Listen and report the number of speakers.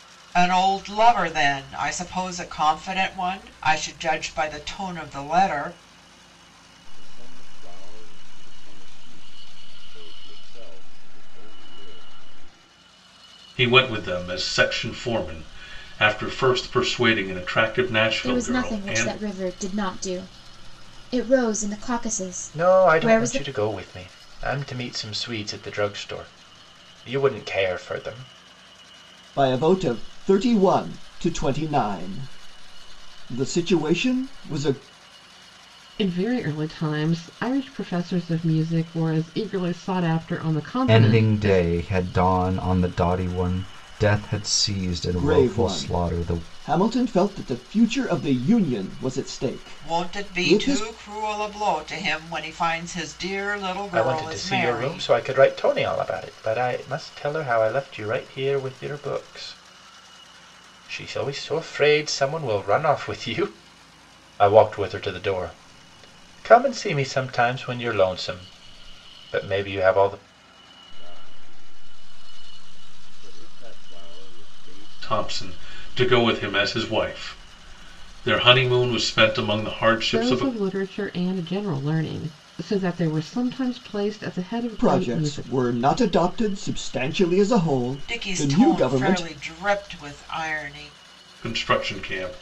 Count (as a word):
eight